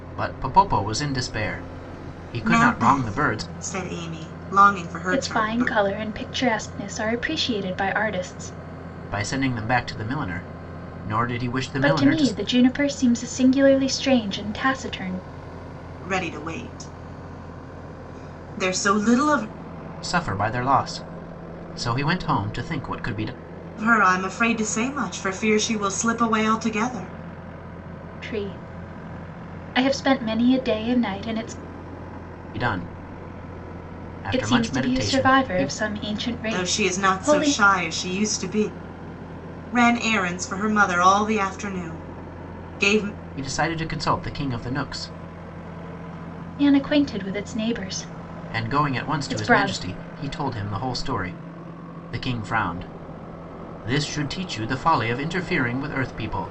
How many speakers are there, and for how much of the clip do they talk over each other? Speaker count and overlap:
3, about 11%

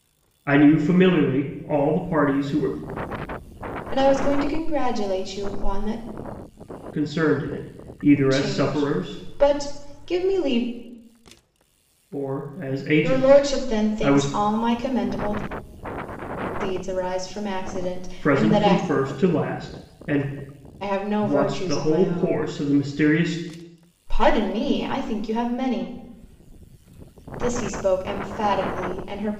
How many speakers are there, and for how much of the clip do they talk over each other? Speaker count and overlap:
2, about 14%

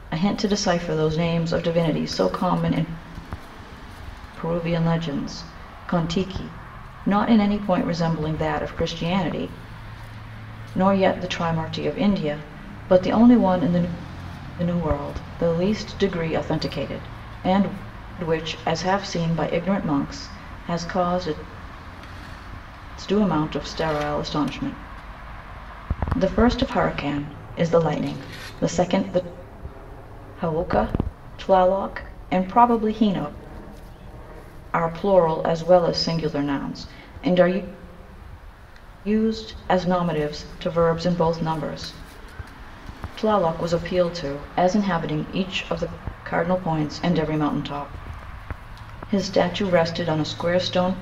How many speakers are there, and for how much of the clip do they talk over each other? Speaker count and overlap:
1, no overlap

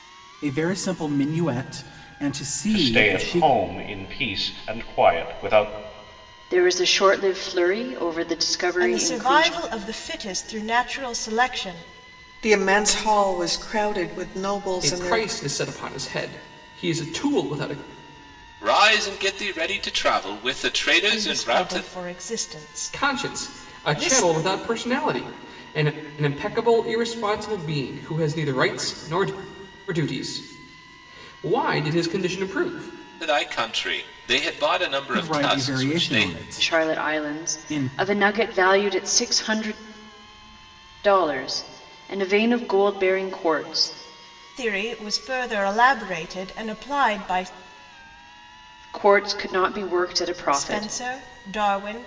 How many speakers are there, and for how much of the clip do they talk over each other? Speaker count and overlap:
7, about 14%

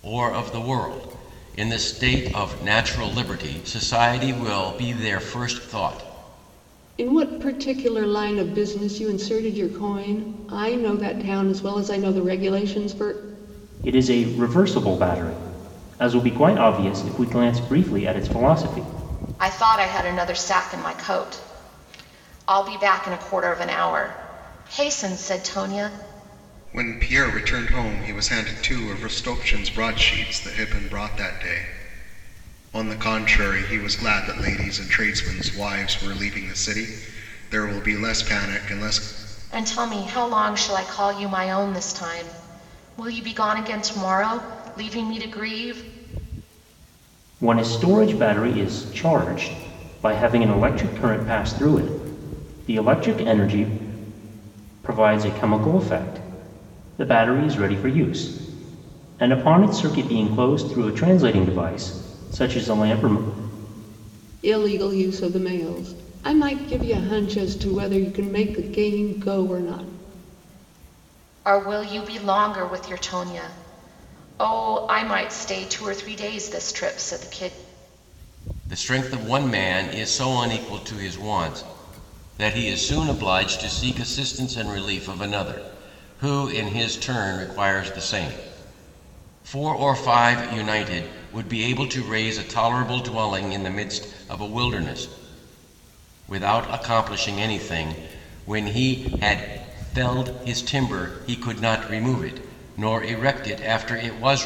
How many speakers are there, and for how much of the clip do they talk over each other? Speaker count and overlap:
5, no overlap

